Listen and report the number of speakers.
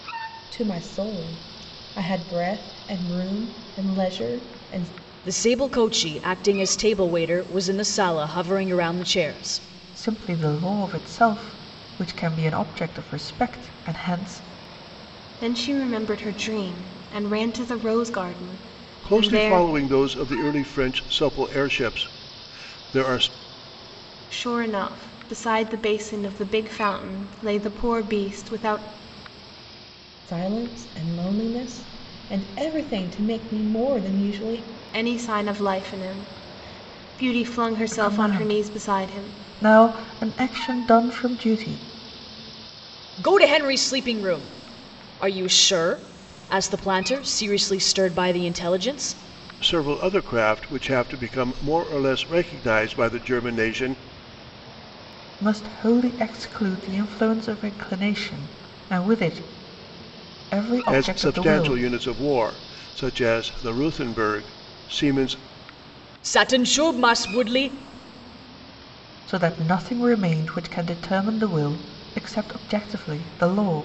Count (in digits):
5